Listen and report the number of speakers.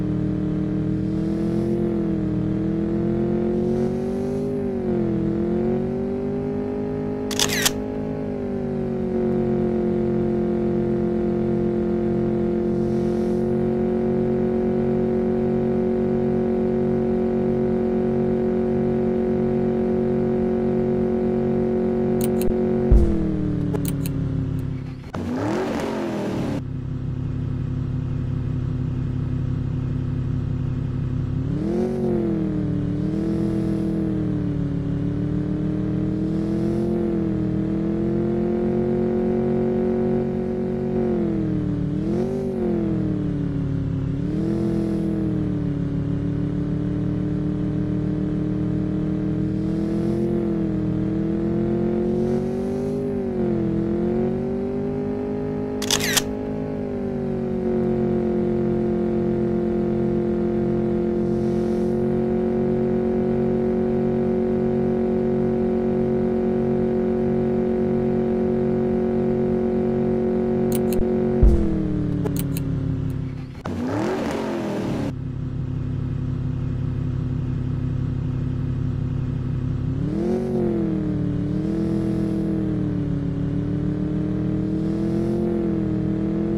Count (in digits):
0